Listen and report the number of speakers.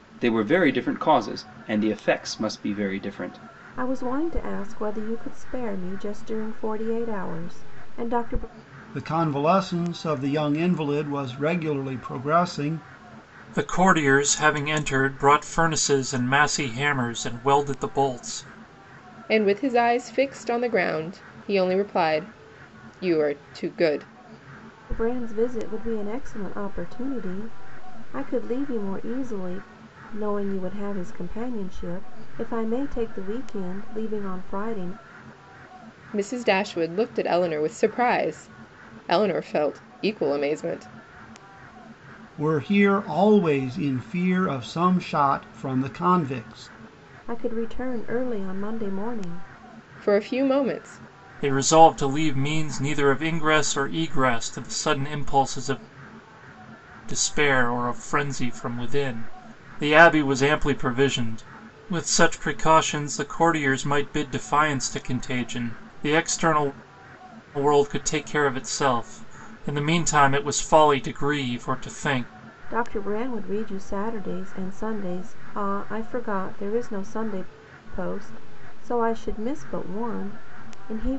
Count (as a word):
five